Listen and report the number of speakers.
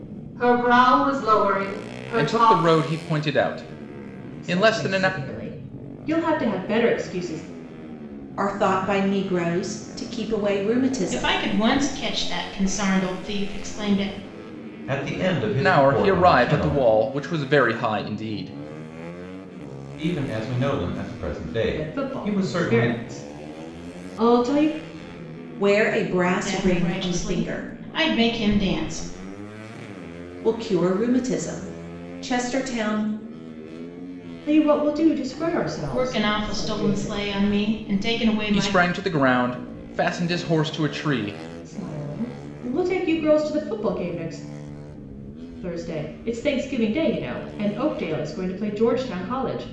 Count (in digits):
6